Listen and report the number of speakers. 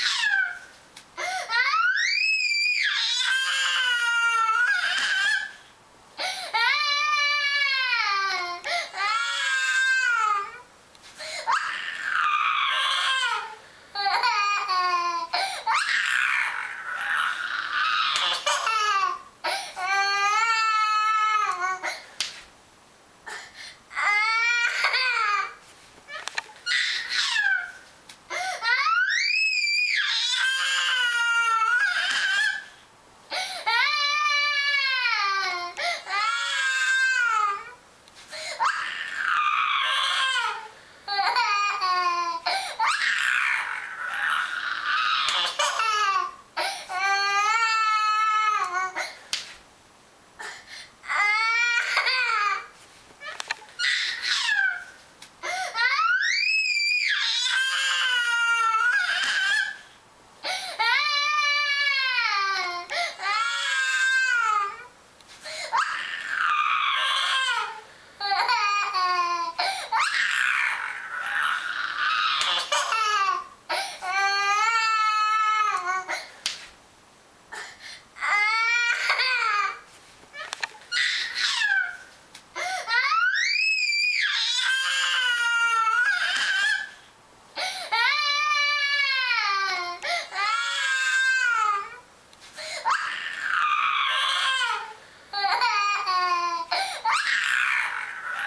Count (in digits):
0